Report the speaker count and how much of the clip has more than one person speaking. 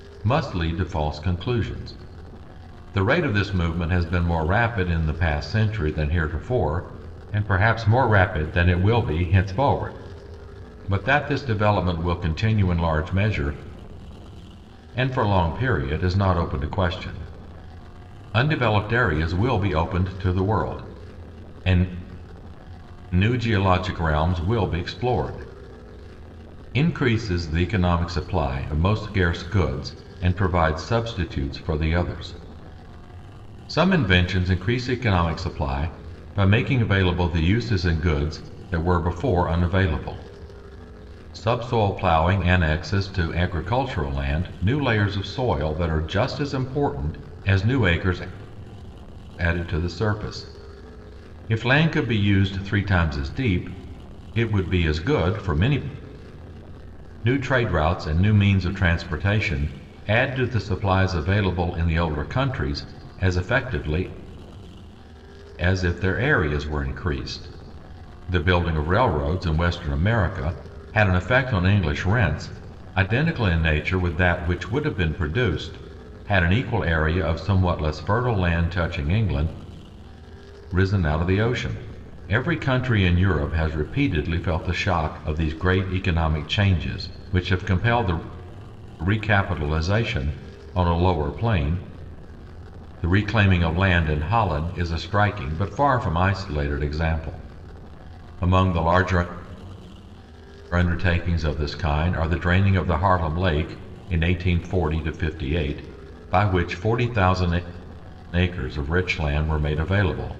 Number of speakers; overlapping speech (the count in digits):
1, no overlap